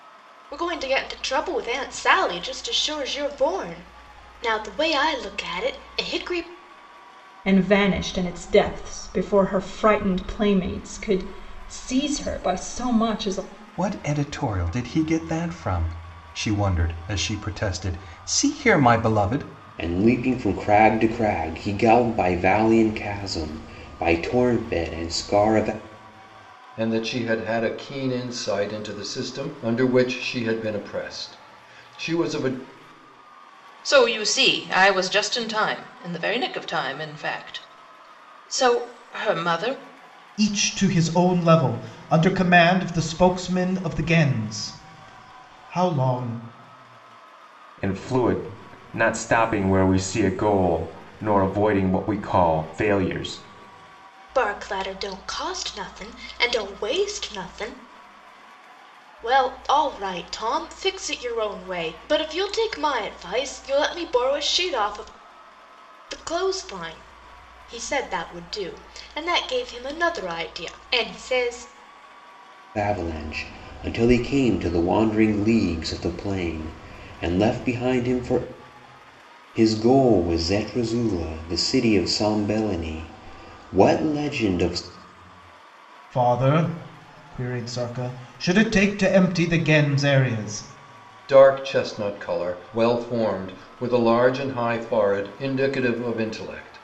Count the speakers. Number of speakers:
eight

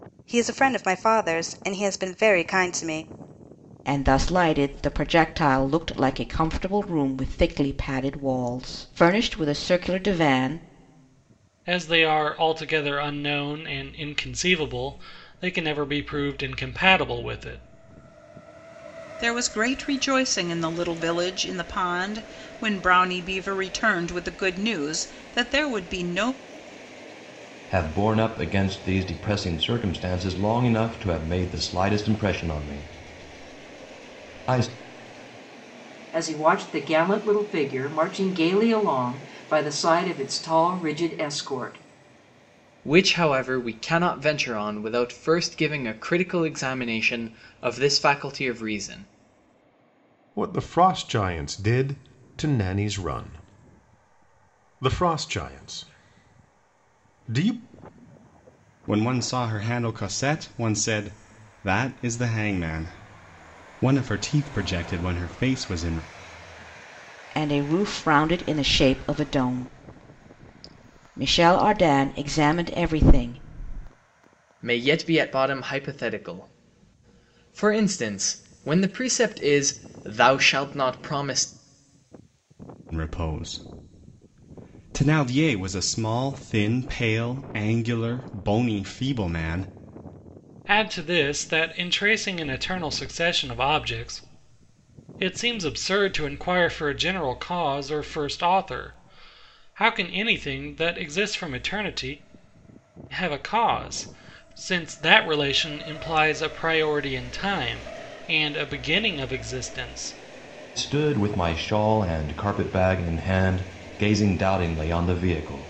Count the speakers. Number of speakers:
nine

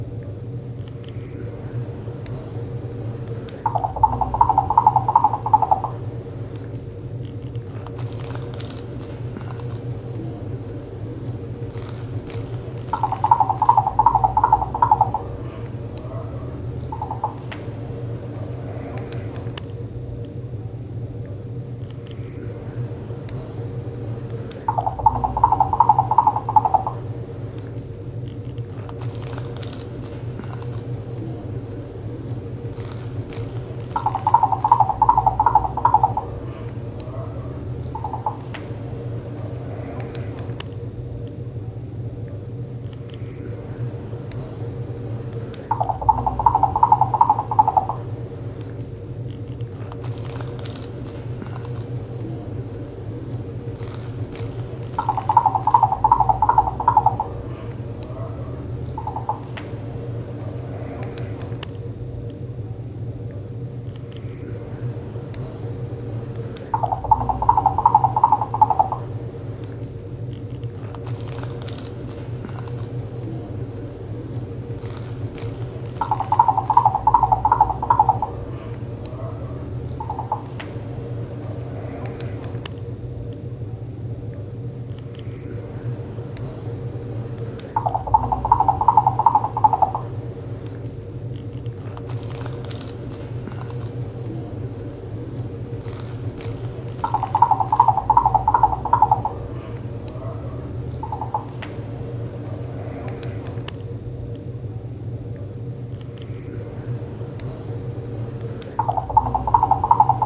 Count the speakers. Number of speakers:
zero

